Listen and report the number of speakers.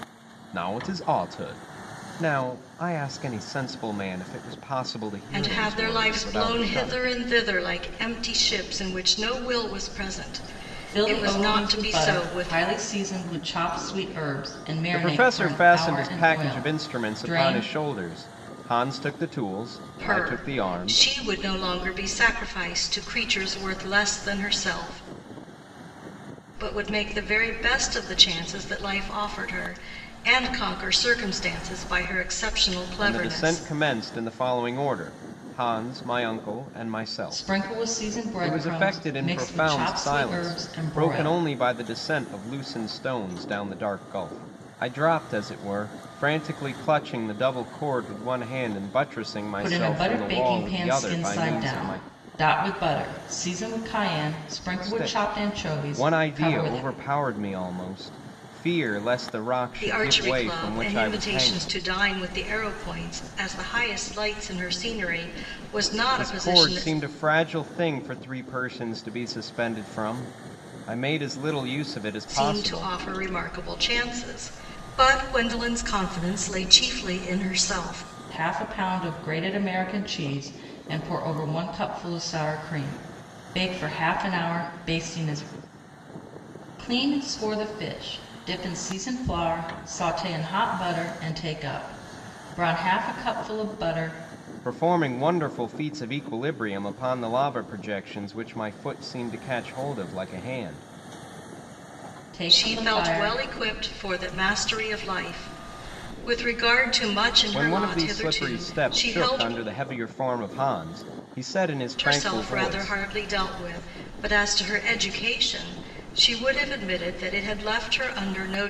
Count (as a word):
three